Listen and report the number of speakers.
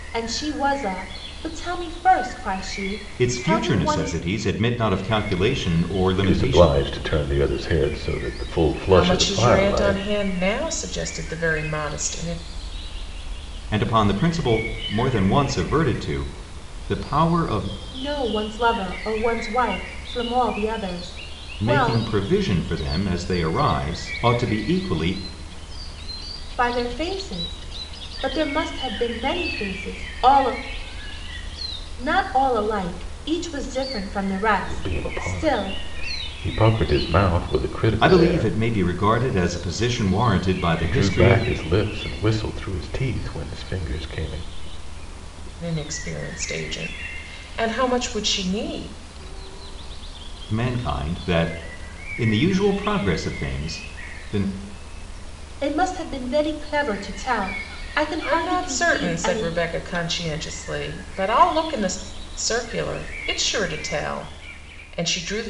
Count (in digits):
4